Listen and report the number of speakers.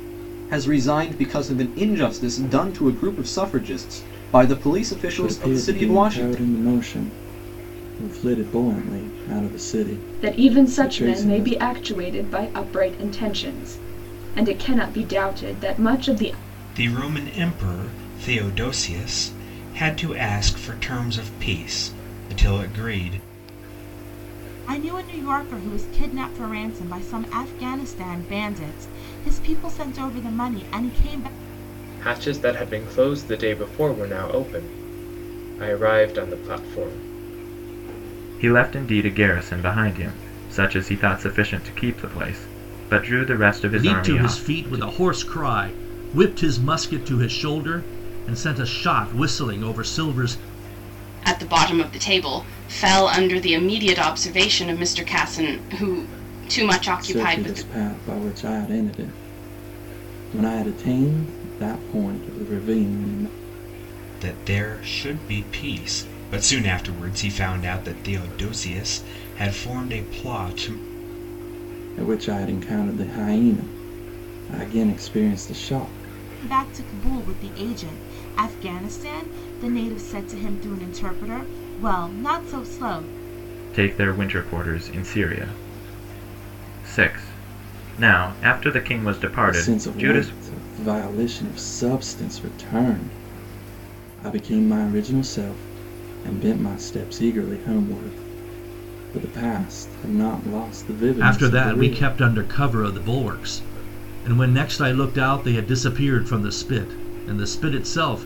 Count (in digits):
9